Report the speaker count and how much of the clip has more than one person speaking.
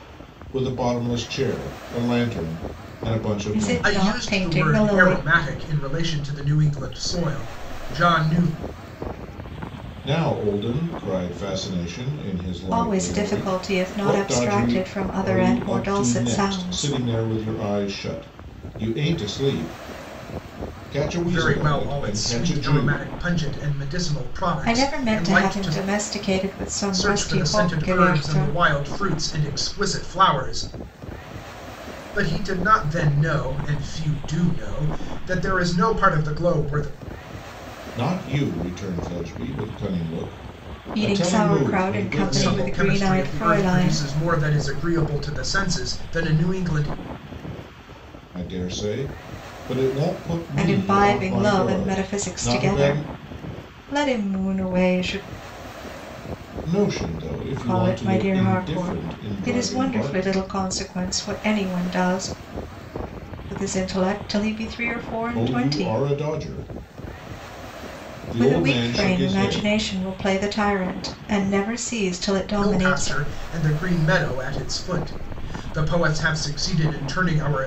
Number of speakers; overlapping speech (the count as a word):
three, about 27%